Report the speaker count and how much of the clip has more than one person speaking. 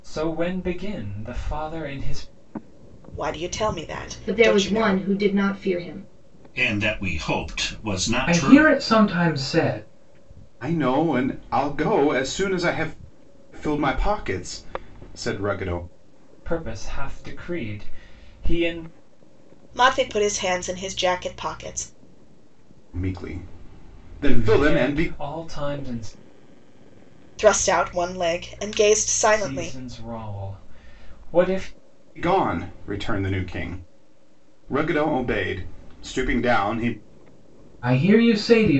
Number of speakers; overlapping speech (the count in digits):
6, about 7%